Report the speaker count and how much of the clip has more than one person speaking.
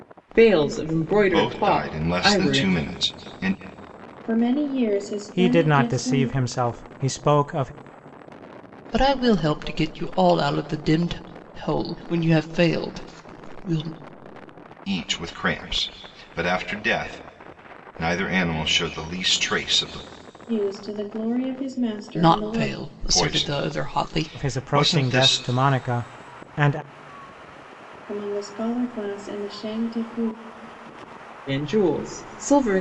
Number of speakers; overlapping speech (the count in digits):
5, about 17%